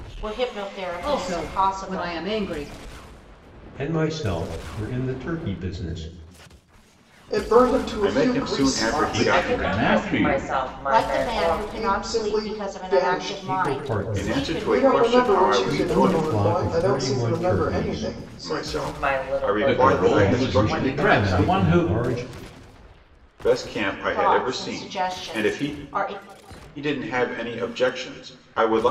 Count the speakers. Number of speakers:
7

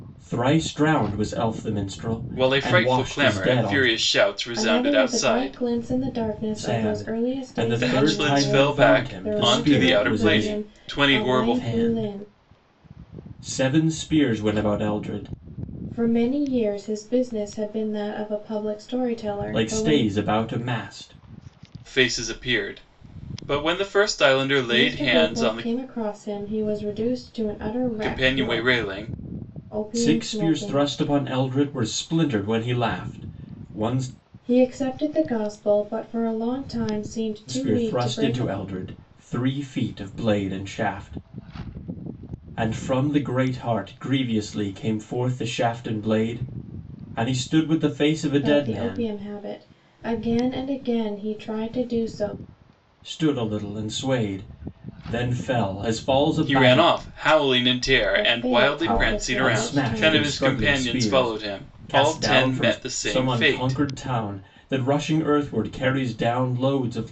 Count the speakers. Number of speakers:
3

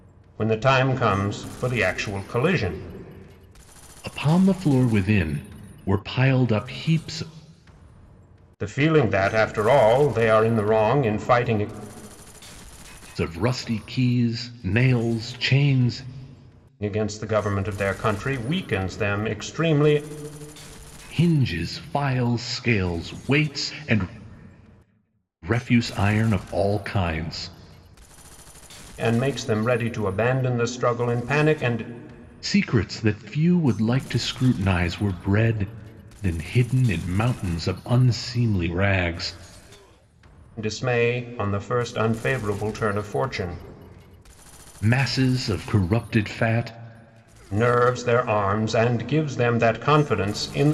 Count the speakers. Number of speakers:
2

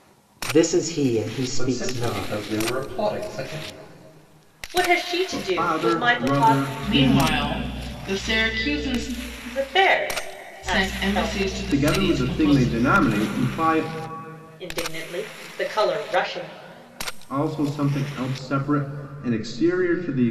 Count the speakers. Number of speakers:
5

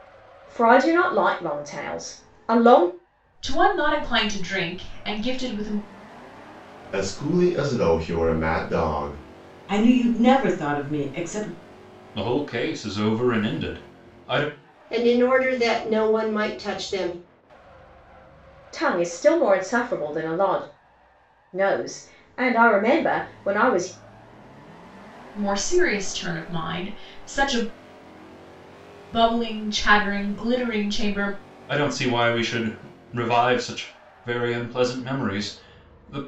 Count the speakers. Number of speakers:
6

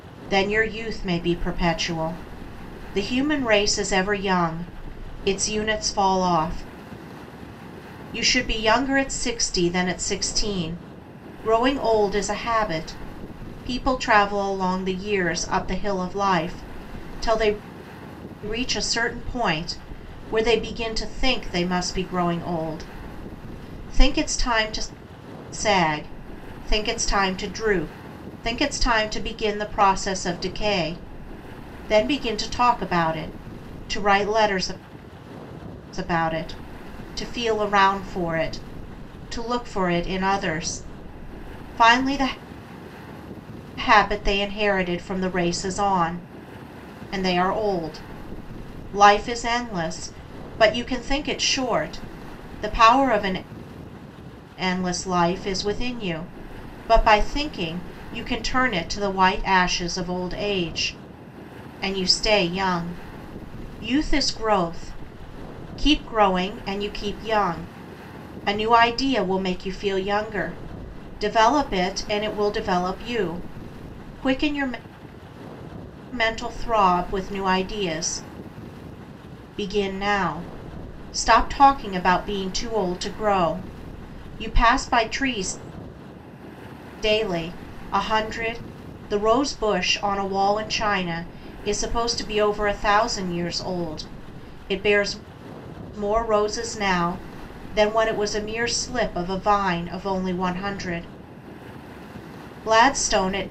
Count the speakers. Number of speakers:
1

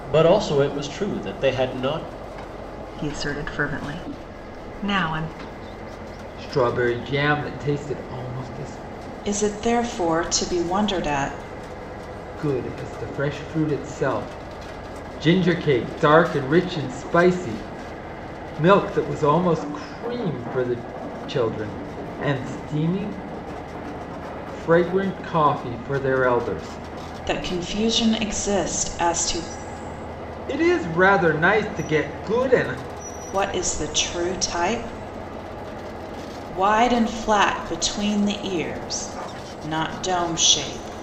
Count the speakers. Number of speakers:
4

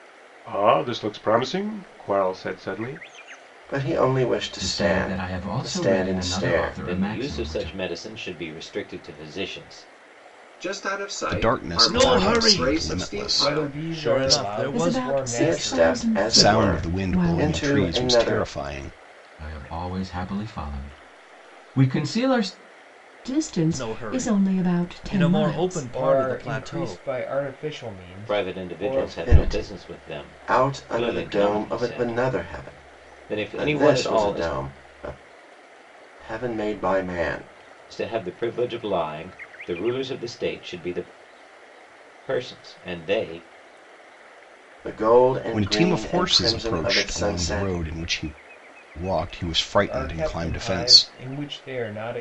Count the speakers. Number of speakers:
9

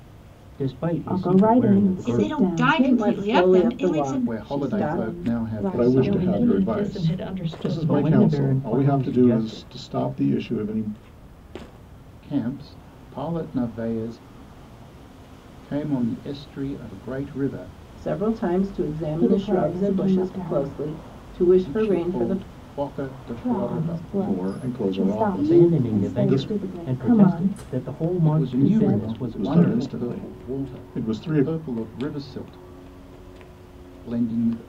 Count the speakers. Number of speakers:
8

